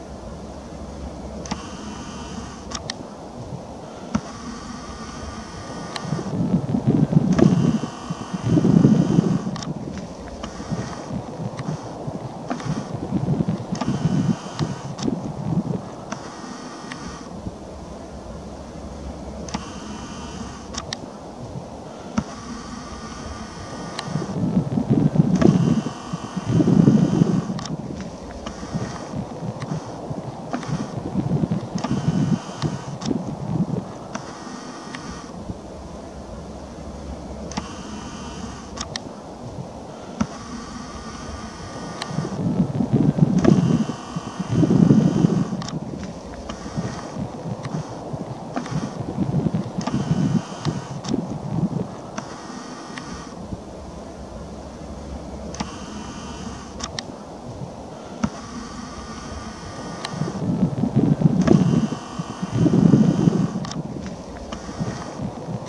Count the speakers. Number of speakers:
zero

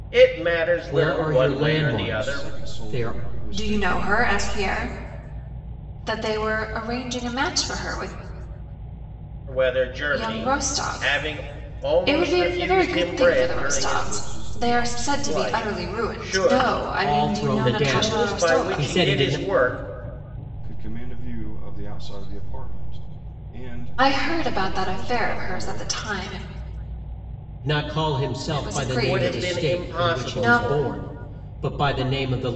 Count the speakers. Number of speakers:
four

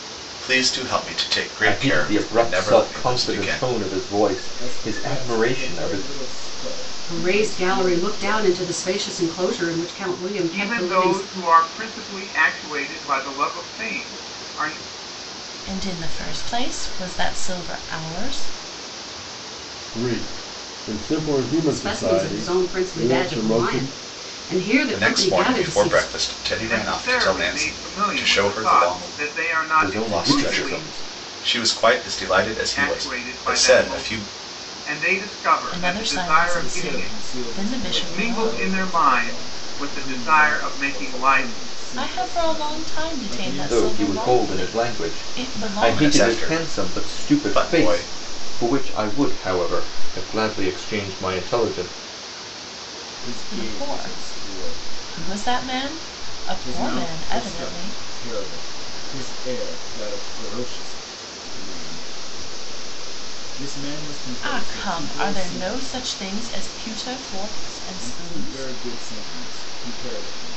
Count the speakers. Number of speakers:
seven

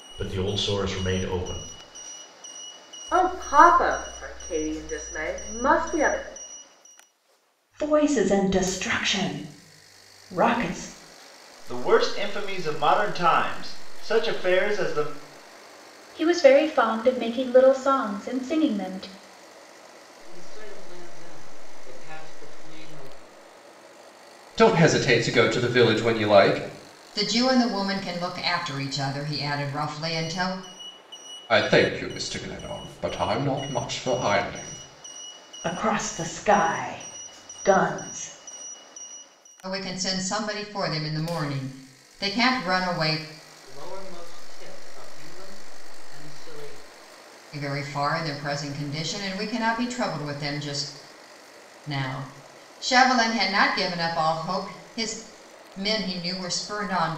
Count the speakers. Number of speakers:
eight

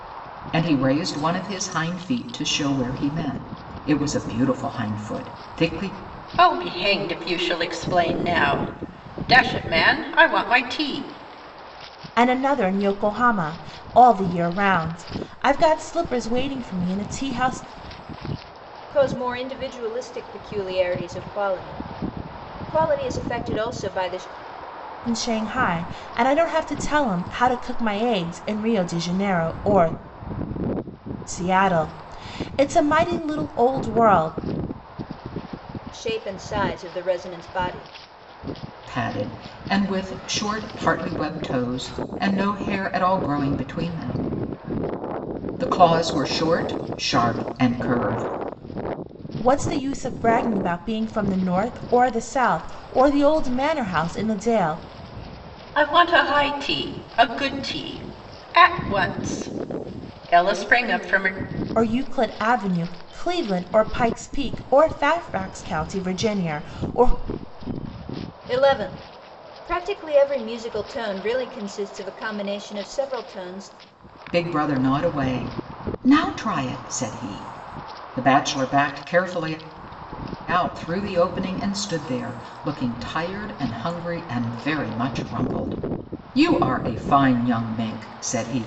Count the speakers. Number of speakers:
four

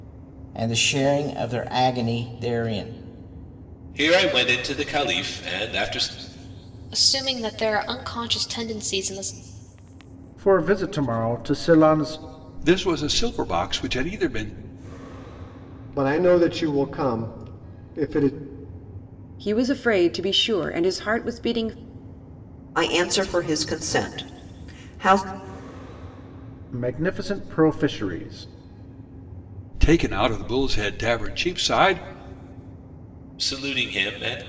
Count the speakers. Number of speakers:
eight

